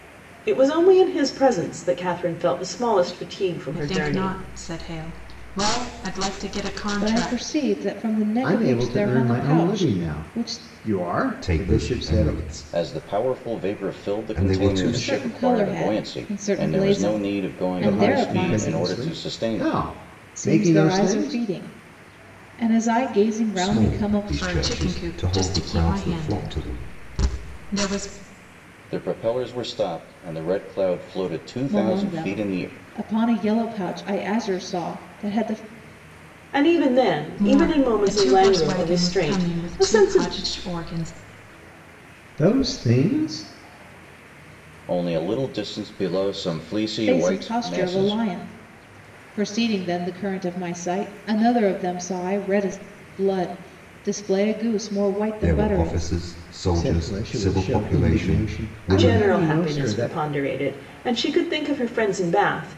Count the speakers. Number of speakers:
6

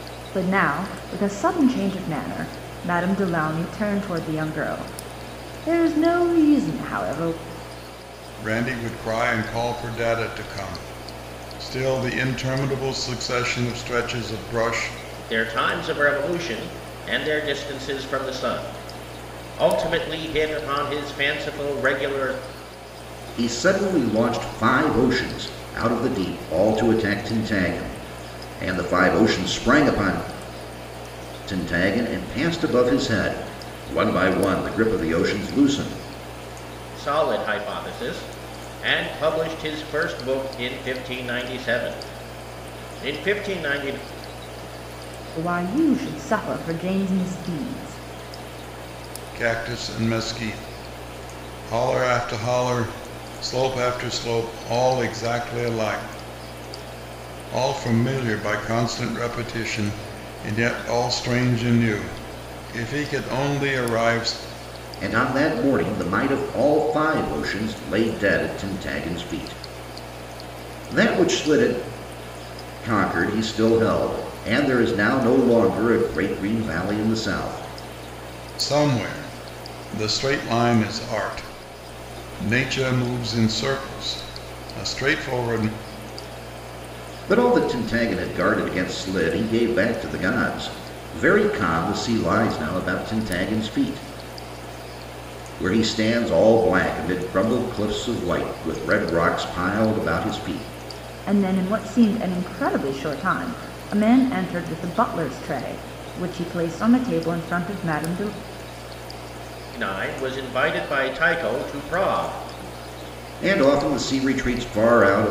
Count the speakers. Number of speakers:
4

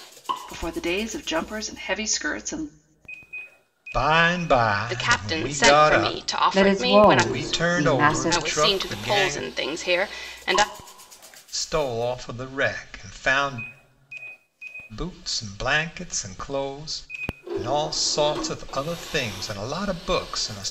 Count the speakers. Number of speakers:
4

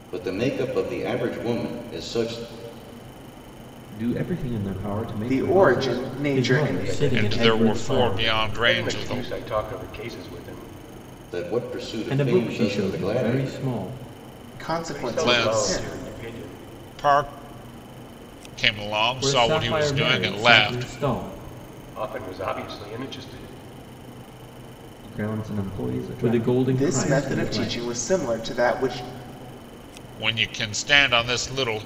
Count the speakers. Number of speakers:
6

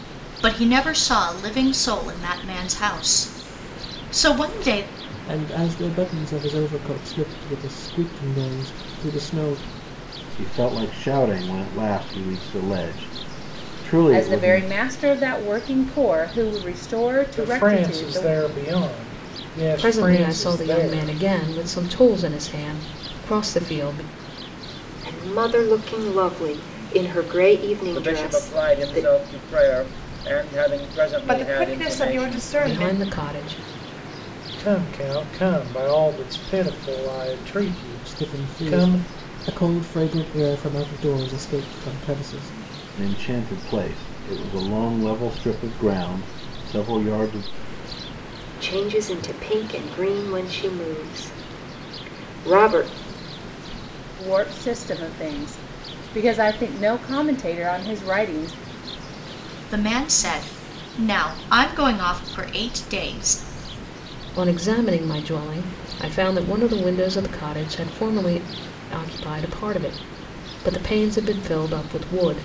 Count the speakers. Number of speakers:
9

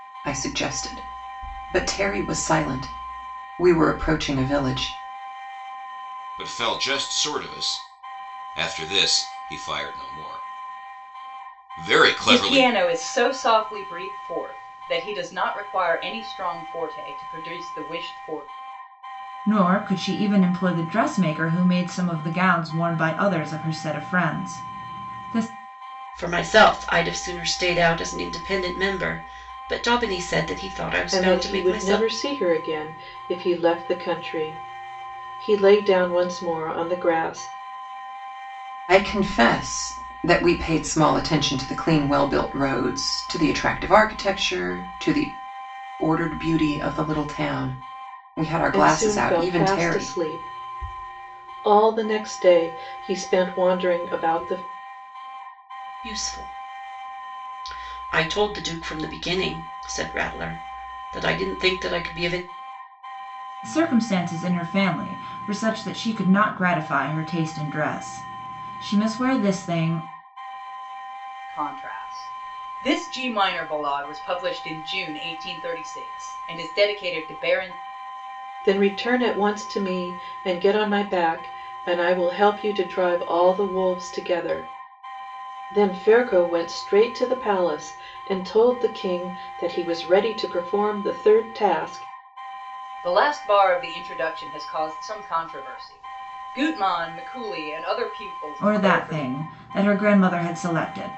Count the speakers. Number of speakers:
6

